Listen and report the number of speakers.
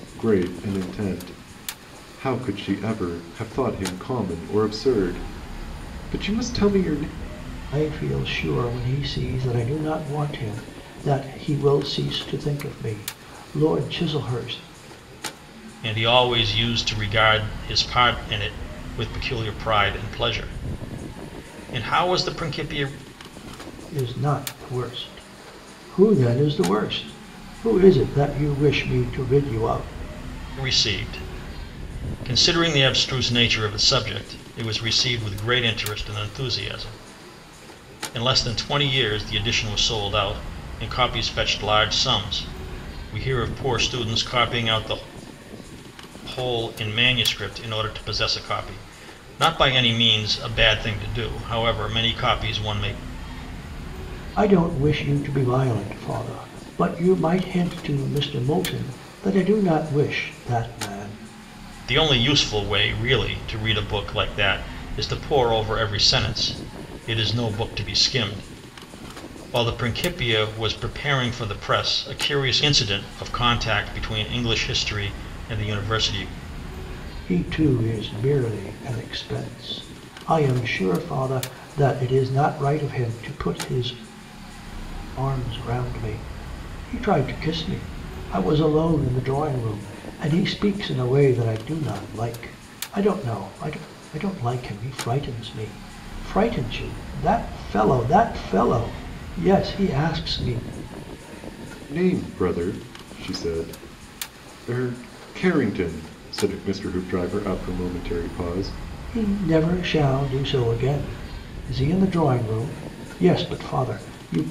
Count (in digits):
3